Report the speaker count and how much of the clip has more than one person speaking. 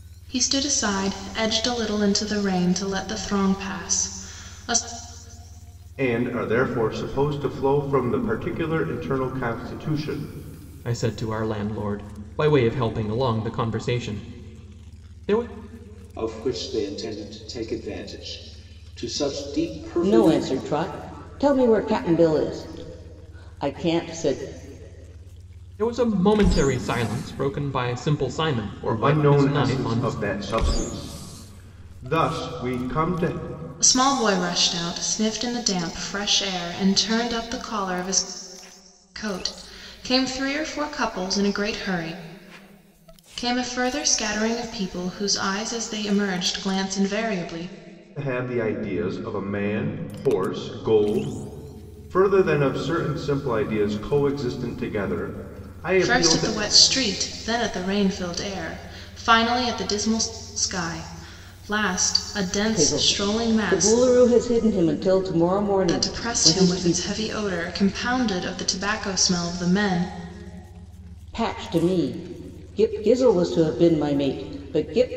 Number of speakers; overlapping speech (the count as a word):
five, about 7%